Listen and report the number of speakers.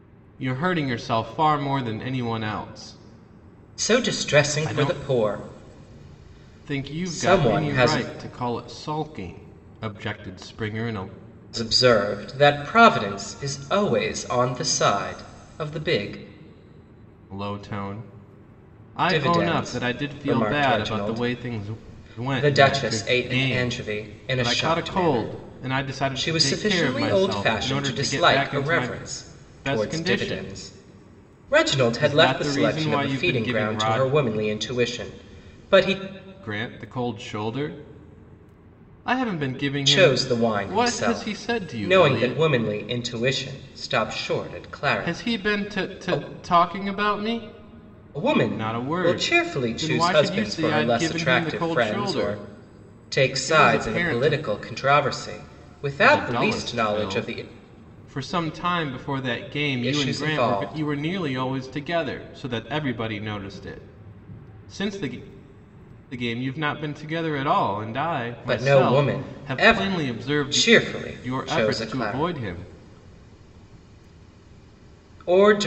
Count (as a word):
two